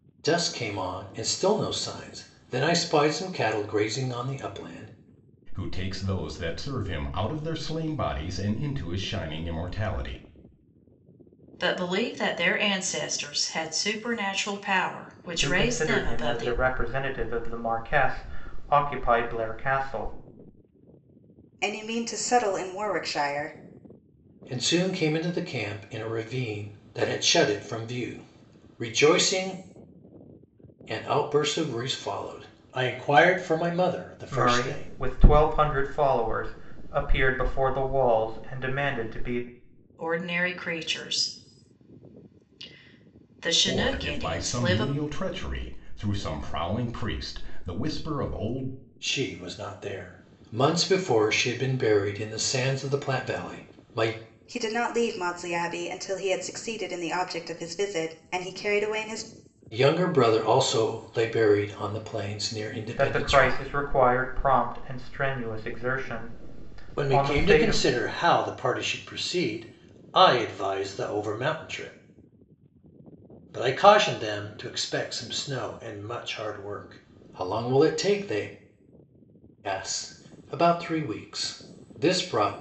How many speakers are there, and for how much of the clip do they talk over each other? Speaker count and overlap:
five, about 6%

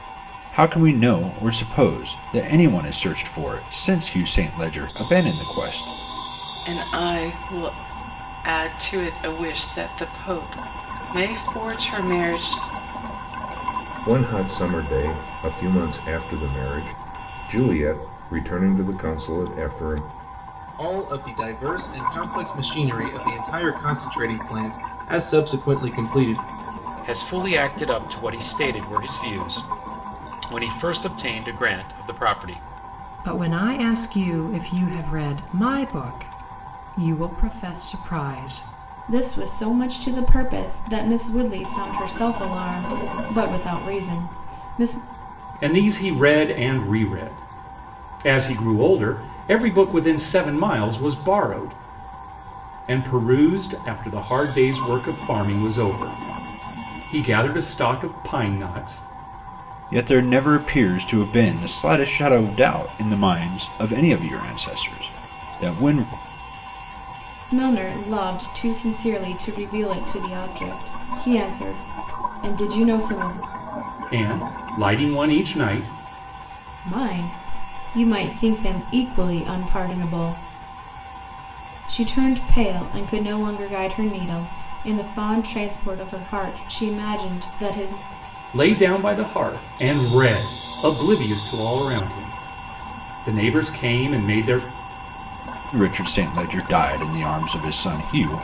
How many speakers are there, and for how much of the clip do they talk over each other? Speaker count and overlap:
eight, no overlap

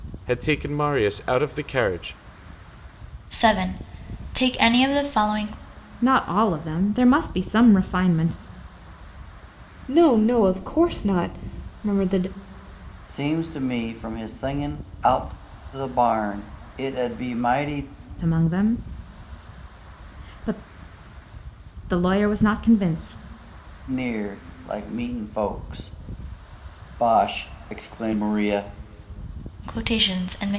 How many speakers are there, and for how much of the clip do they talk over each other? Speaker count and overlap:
five, no overlap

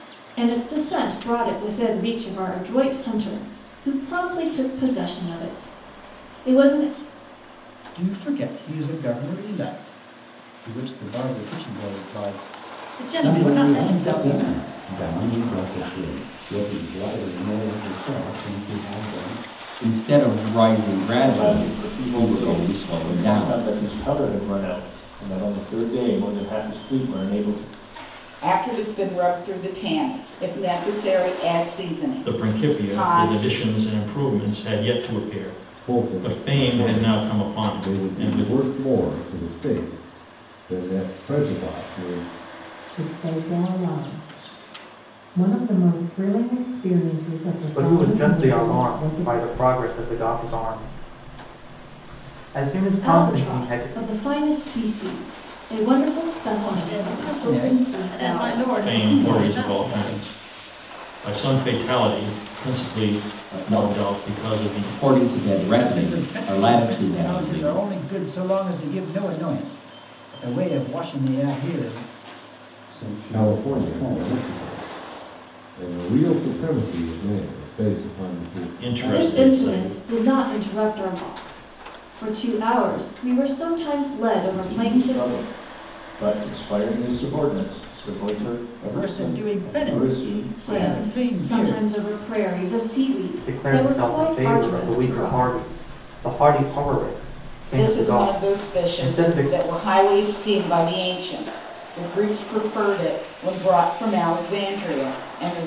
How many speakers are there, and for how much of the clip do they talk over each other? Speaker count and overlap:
ten, about 27%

